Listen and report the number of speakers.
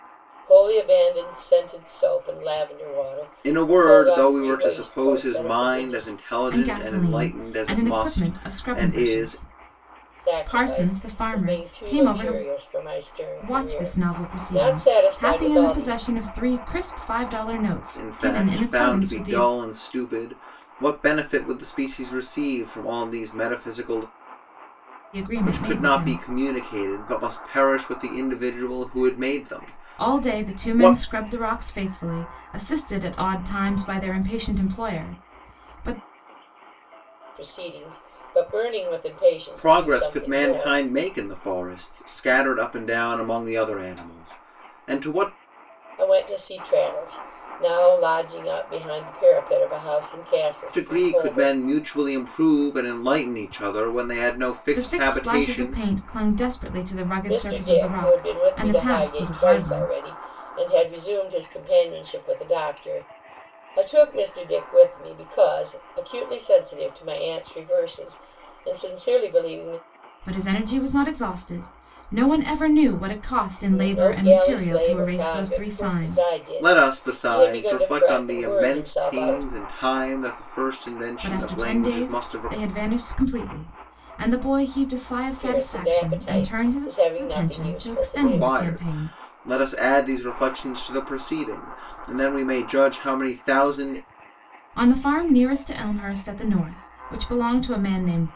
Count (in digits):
3